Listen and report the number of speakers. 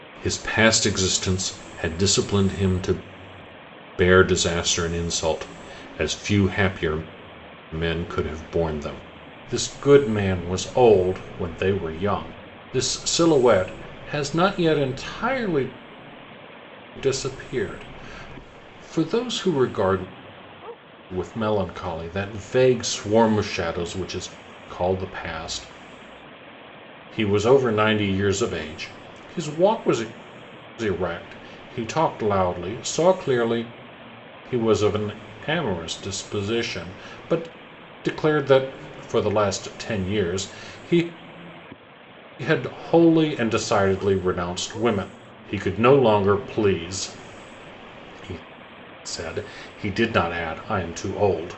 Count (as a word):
one